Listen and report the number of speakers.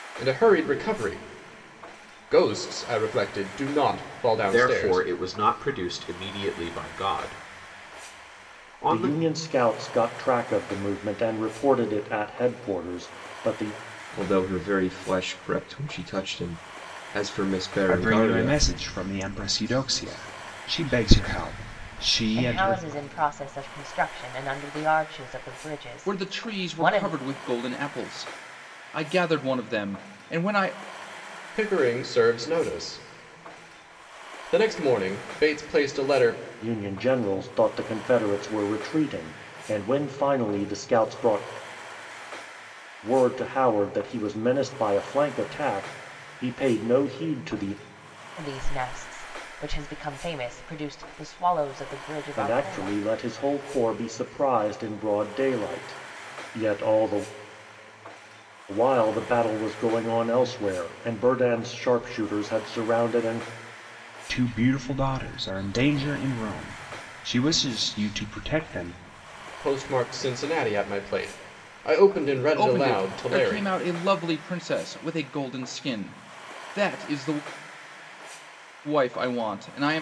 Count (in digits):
7